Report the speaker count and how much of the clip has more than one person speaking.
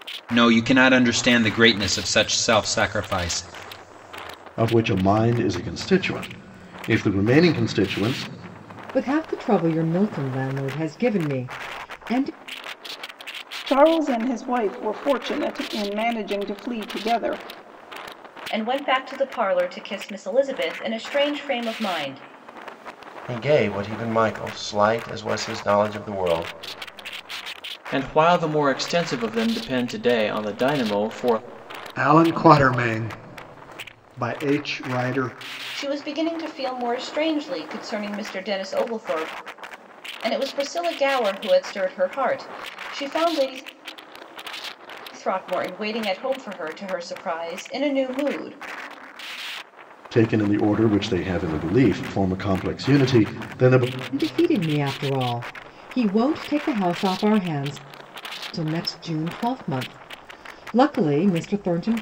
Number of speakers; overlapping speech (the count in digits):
8, no overlap